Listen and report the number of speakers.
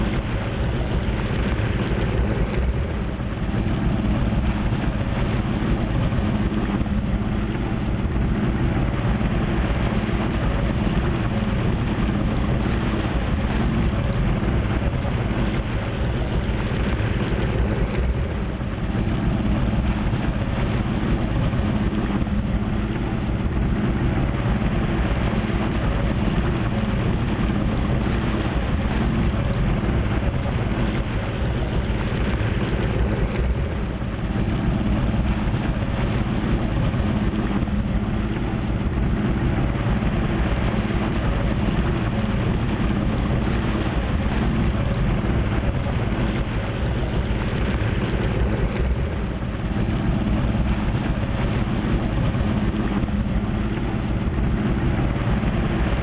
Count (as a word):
zero